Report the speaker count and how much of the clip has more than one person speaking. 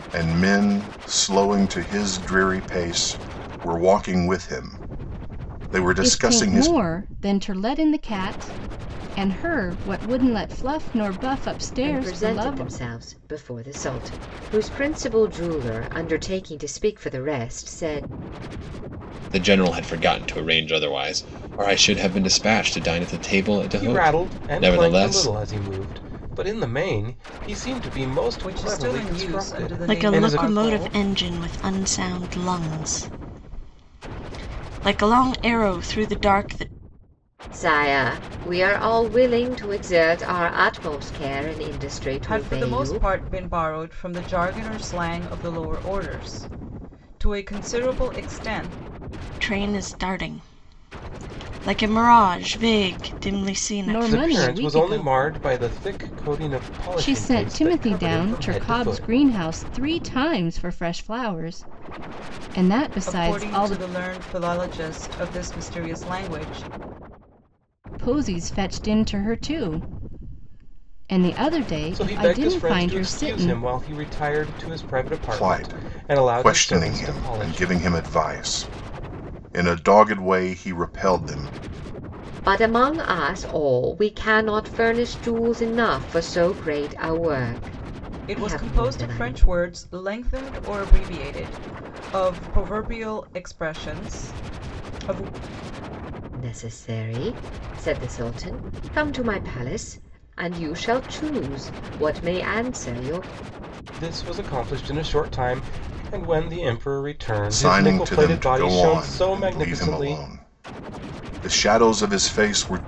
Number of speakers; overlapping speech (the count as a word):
seven, about 17%